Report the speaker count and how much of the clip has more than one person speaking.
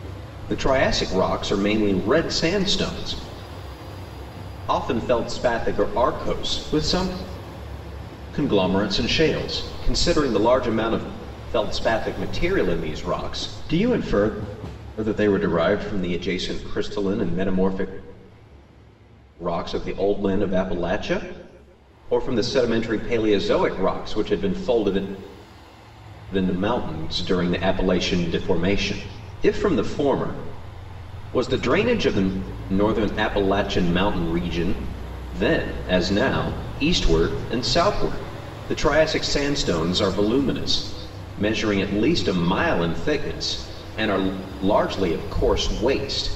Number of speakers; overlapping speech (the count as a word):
one, no overlap